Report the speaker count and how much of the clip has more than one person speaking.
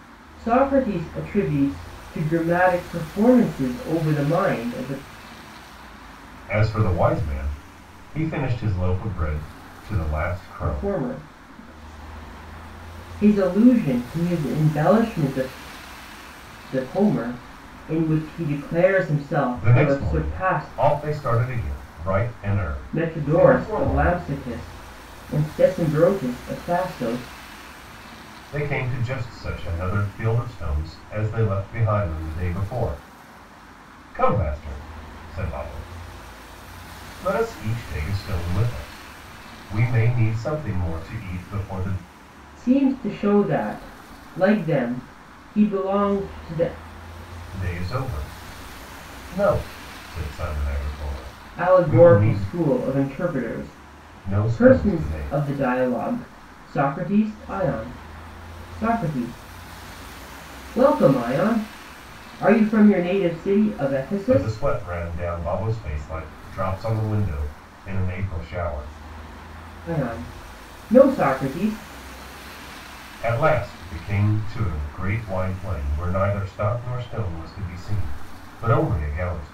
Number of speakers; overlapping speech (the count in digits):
2, about 7%